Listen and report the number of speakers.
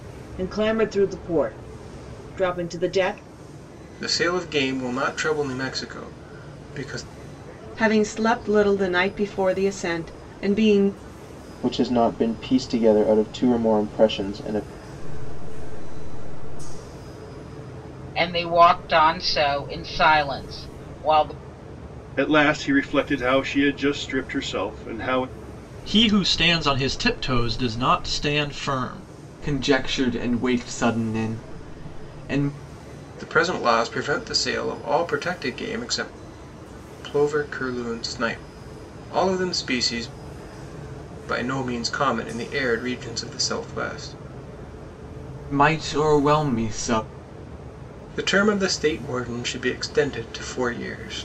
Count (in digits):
9